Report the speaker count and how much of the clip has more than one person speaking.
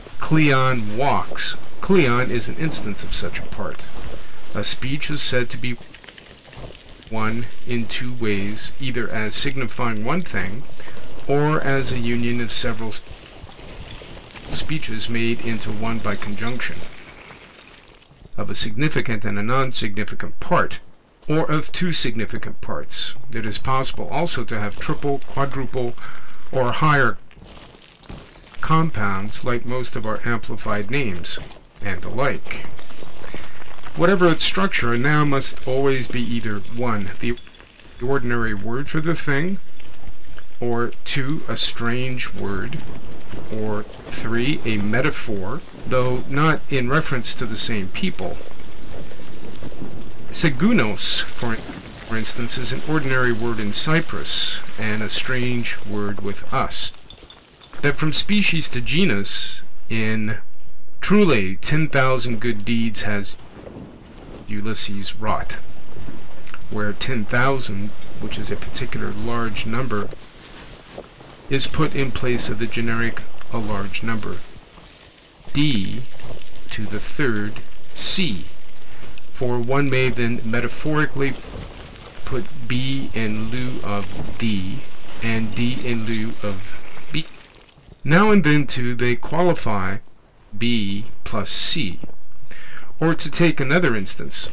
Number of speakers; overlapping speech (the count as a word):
one, no overlap